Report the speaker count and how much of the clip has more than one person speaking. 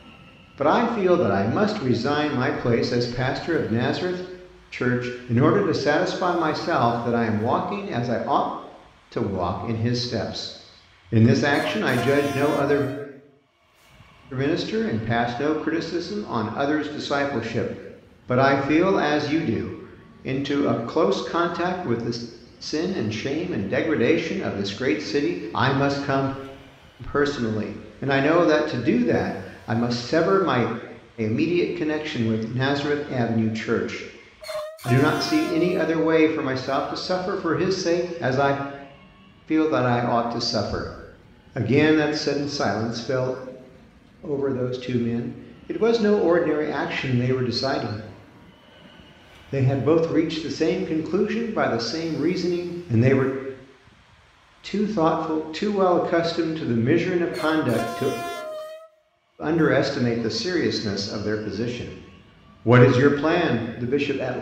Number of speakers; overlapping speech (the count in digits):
1, no overlap